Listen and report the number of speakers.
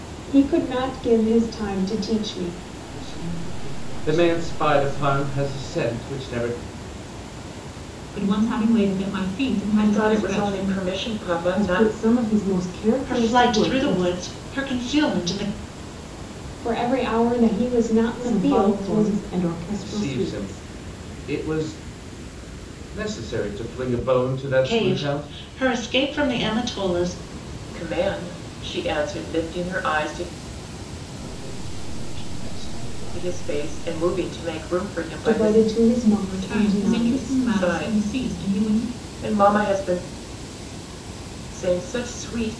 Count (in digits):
7